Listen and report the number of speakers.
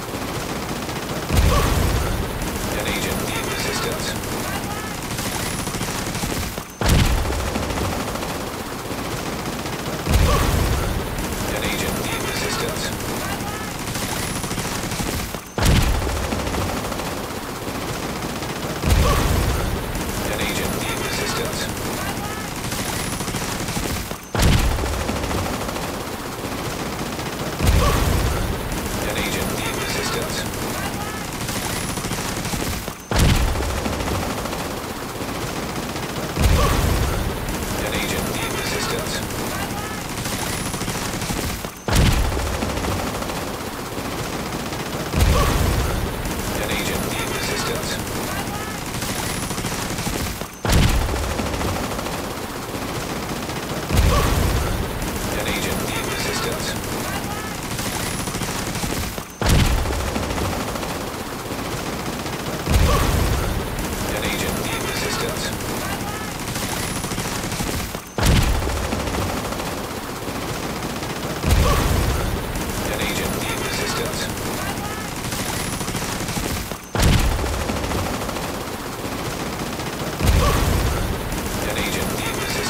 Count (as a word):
zero